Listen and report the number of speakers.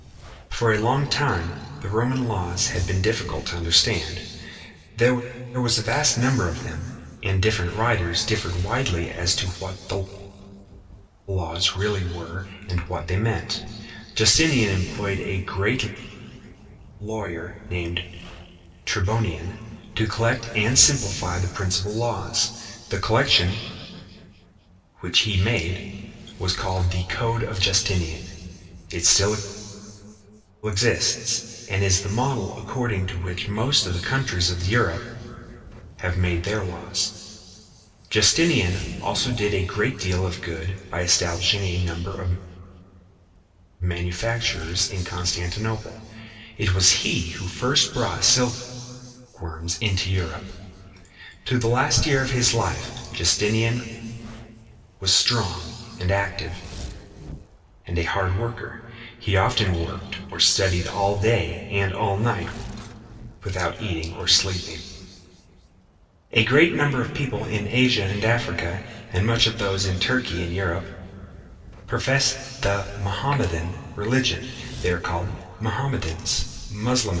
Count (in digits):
1